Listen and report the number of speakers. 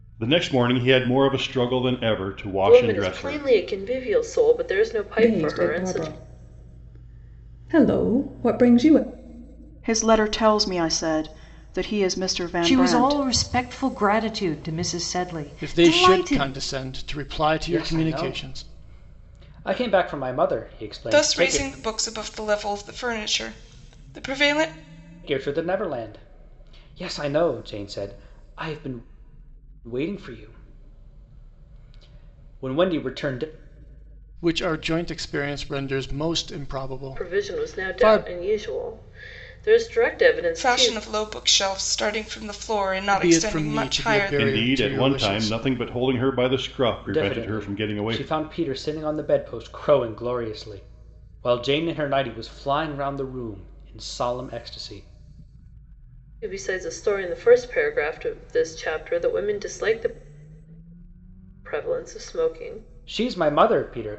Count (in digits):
8